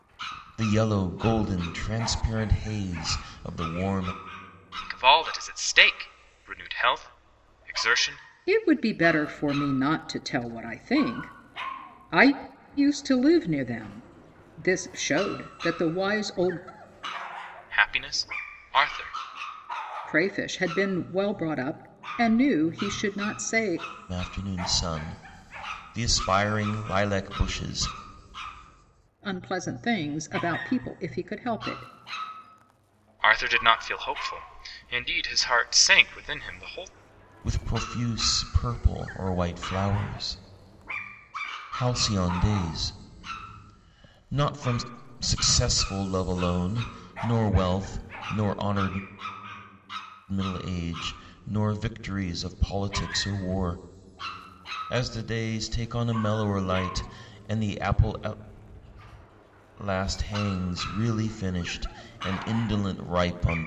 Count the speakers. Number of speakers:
three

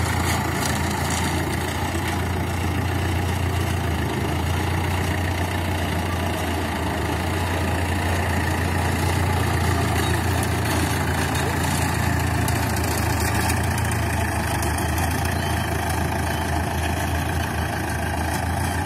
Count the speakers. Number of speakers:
zero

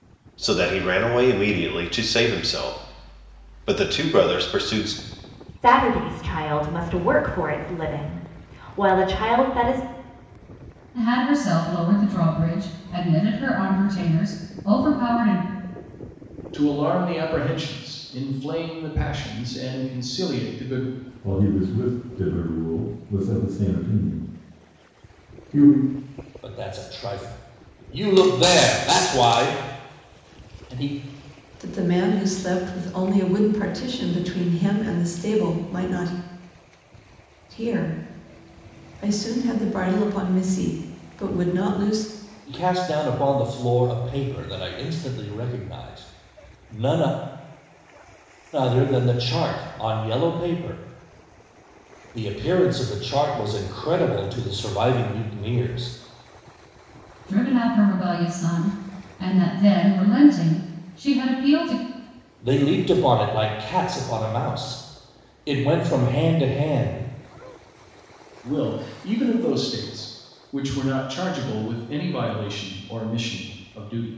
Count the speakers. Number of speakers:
seven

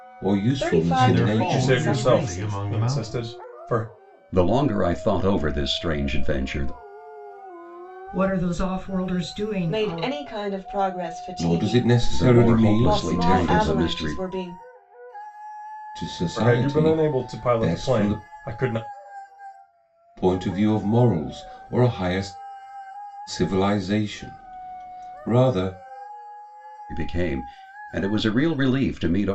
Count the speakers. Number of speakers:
six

